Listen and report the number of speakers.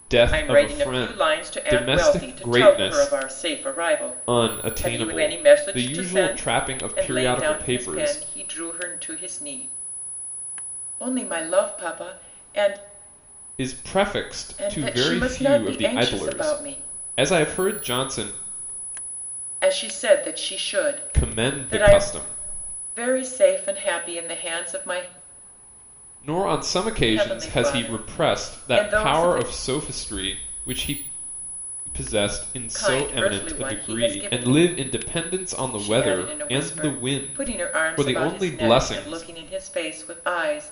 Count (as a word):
two